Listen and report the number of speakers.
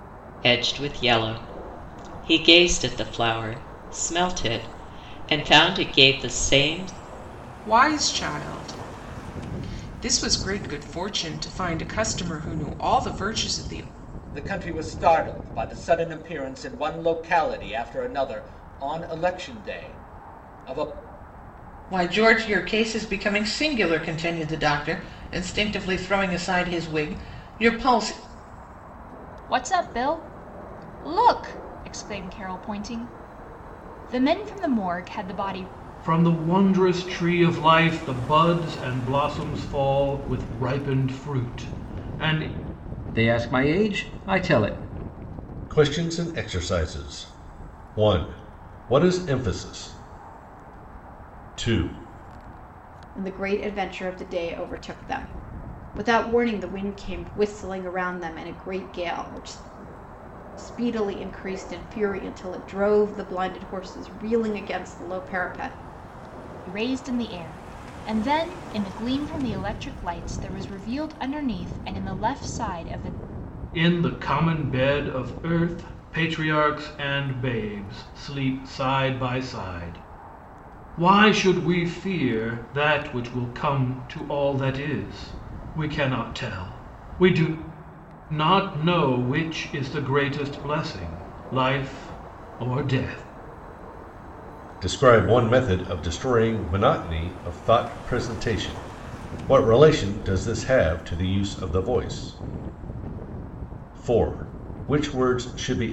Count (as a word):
nine